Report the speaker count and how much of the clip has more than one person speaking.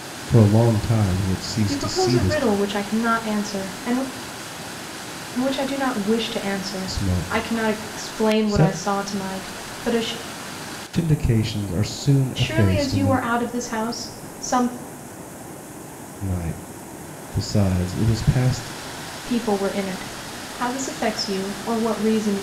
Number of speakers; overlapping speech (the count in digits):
2, about 16%